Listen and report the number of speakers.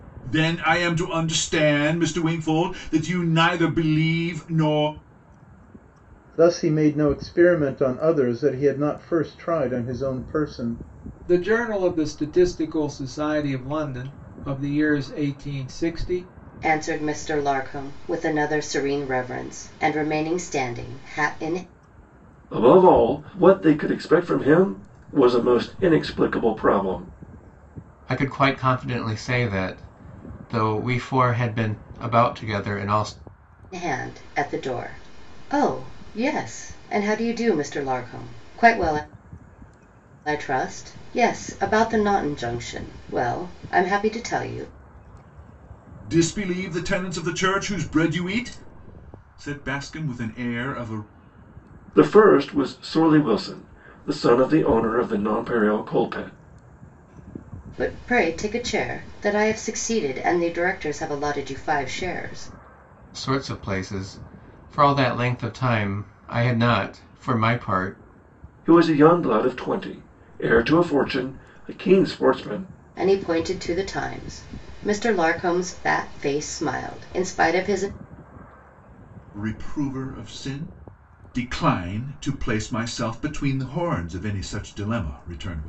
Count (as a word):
six